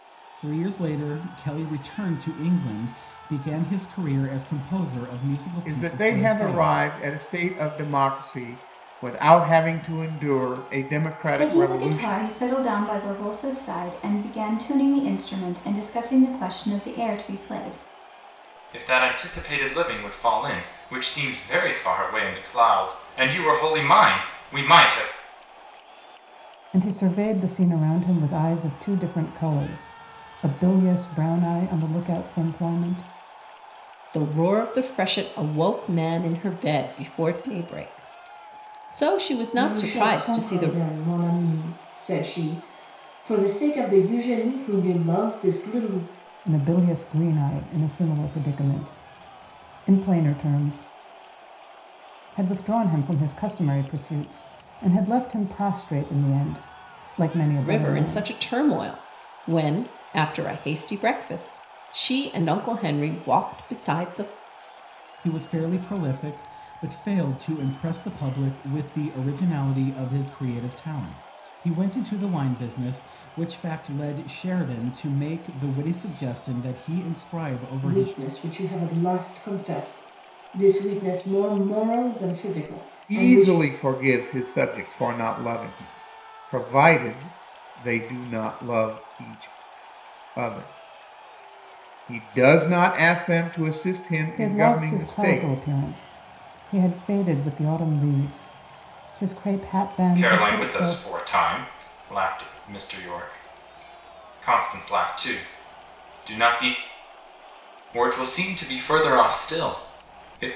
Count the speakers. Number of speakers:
7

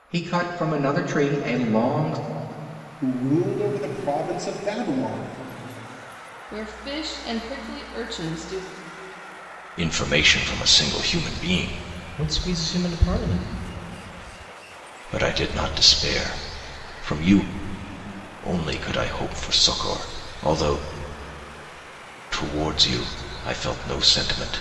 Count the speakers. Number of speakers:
5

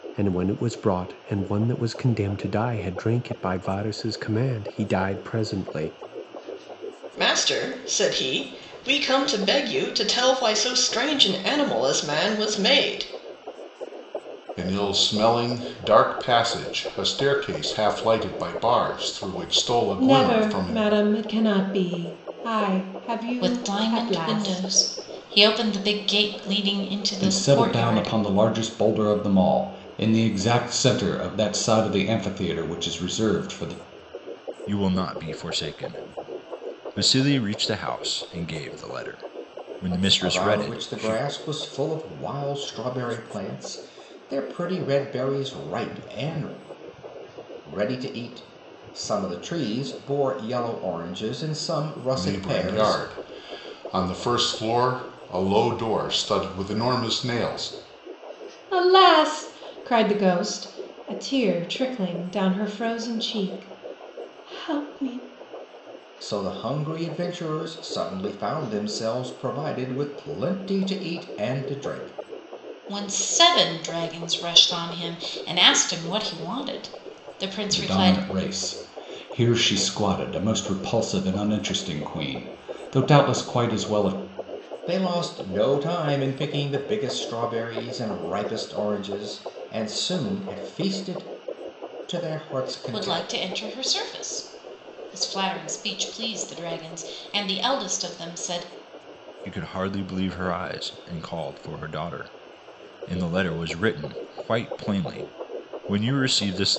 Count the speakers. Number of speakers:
8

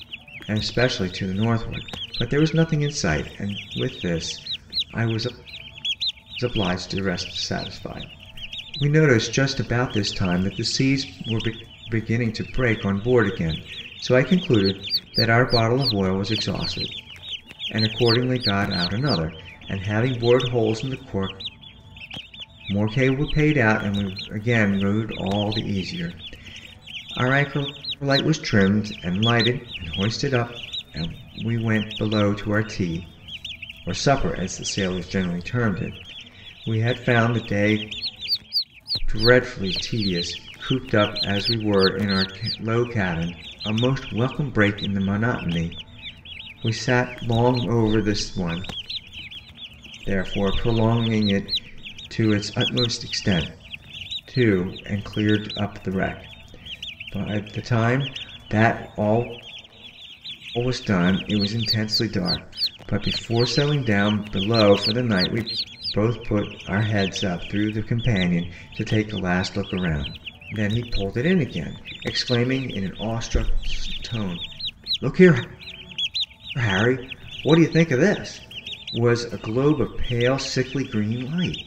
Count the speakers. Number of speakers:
1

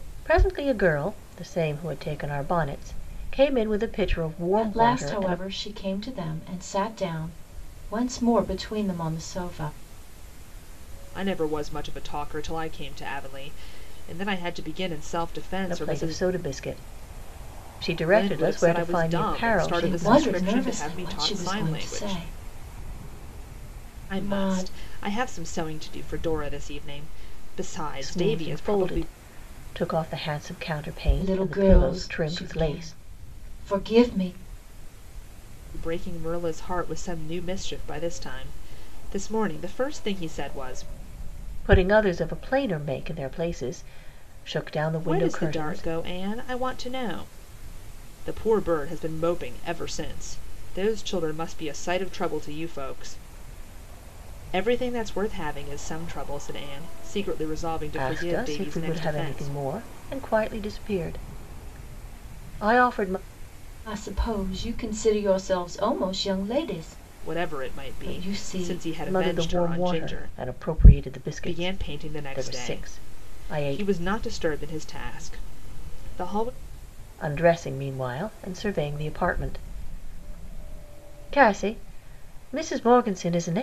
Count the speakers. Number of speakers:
3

